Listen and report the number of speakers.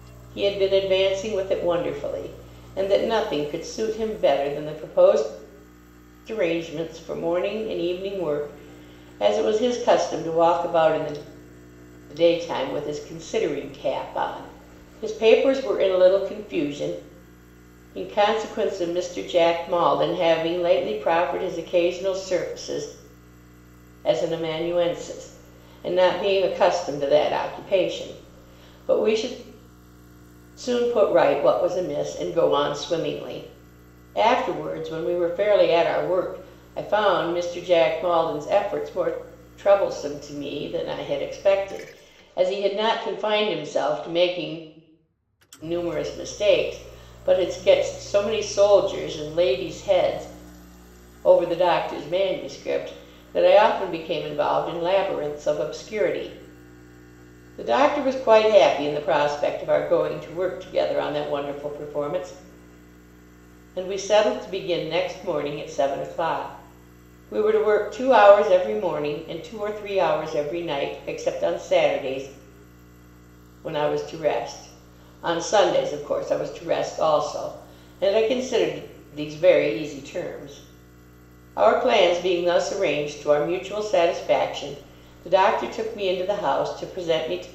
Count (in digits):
1